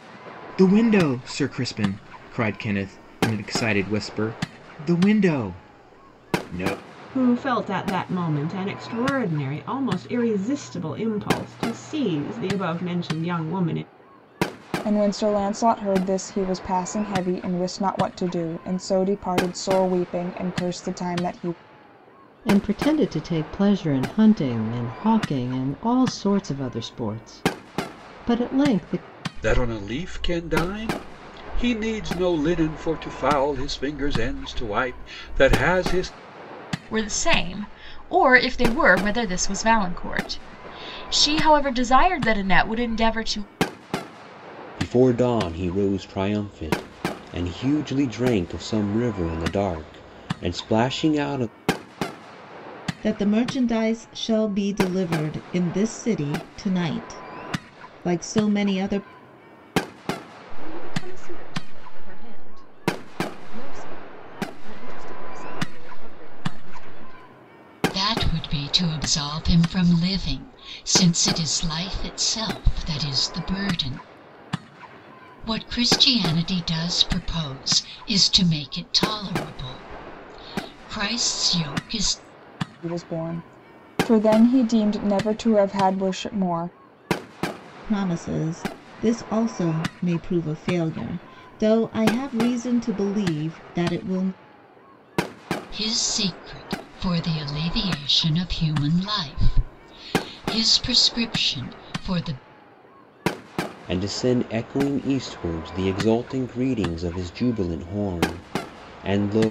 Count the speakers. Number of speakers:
10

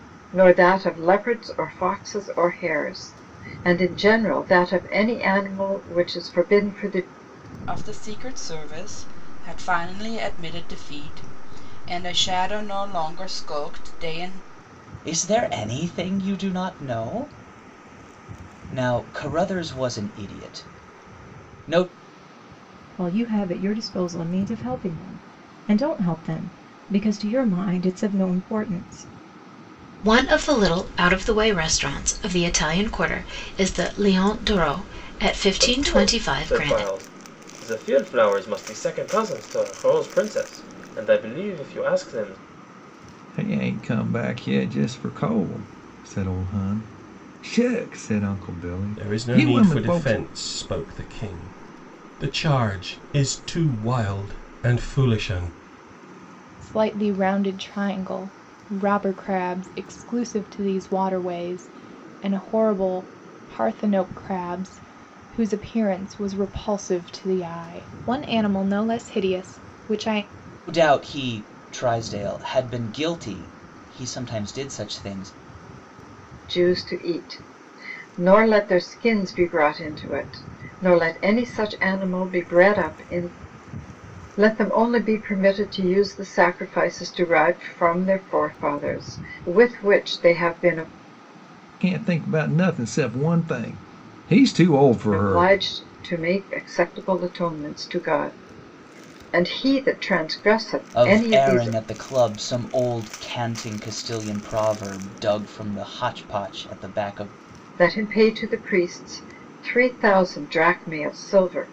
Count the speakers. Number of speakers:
9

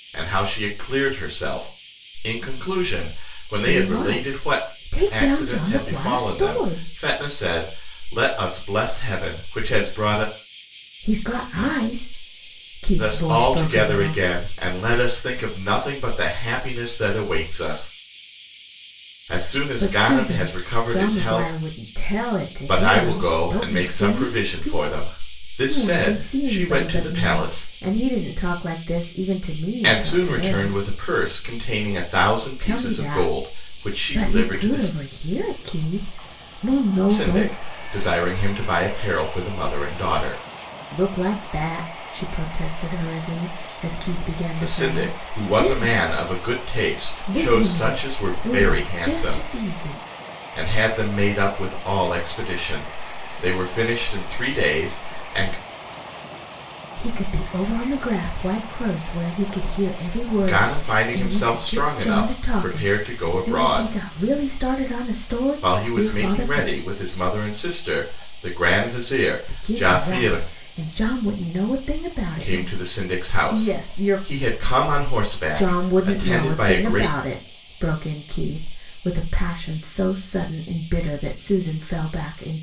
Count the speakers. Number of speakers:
2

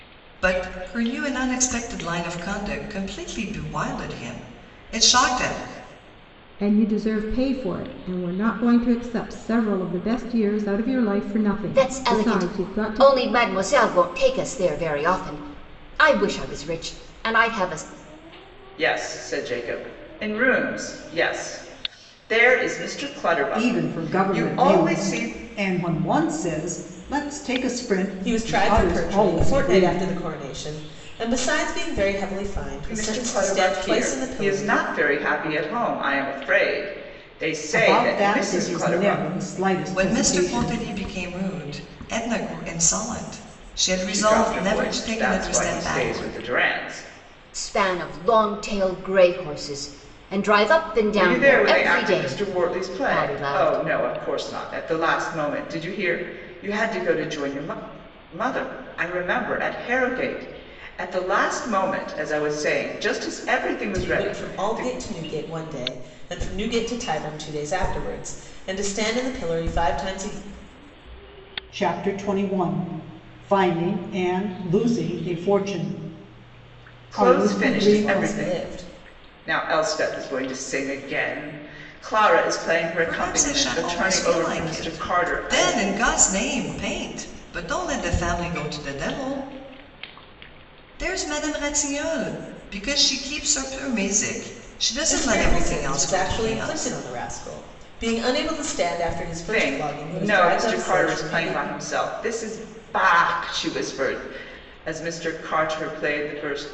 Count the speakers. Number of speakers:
6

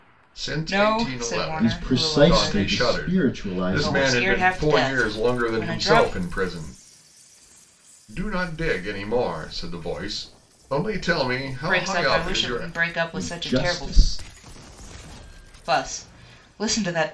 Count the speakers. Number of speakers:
3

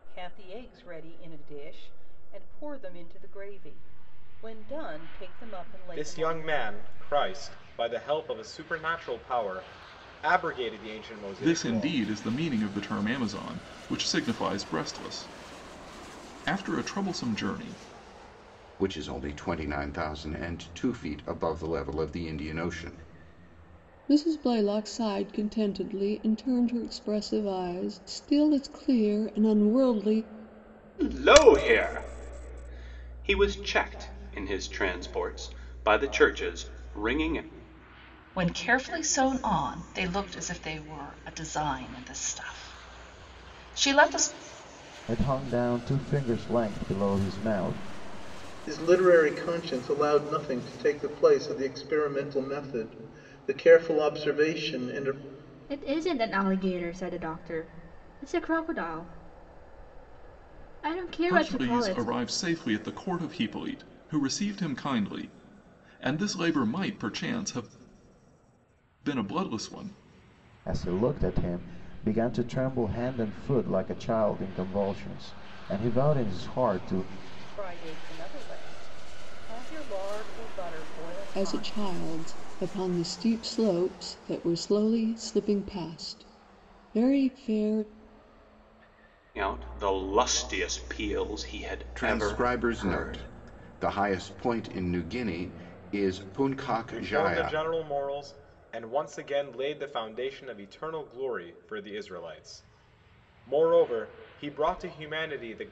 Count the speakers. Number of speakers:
10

